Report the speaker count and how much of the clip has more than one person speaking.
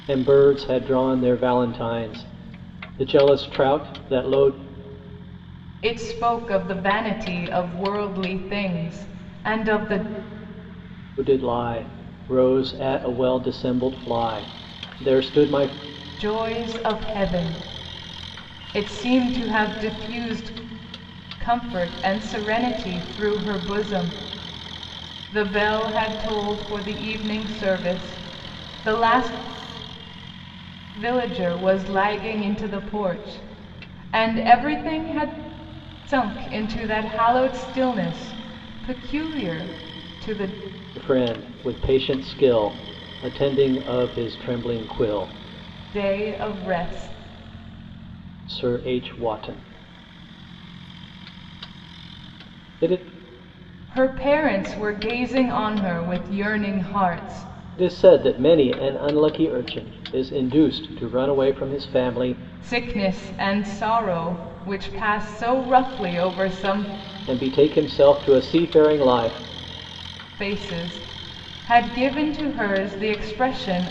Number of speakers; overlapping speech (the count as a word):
two, no overlap